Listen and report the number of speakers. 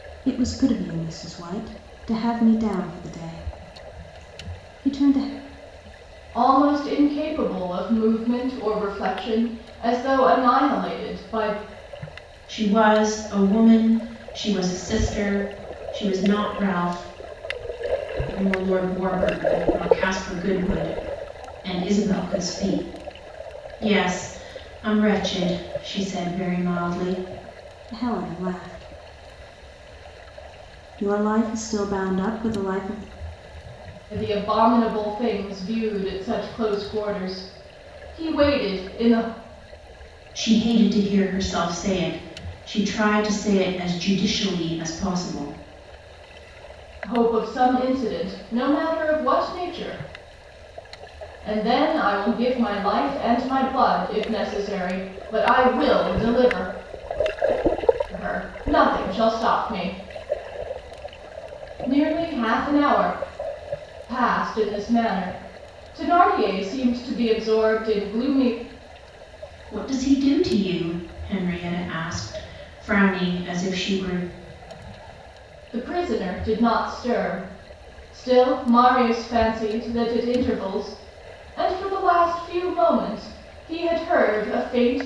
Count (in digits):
3